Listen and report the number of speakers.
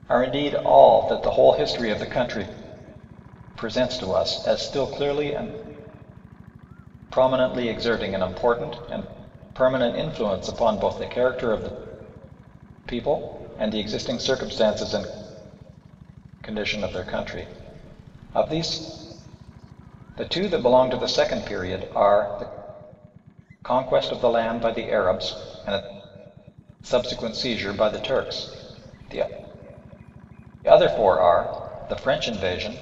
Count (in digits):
1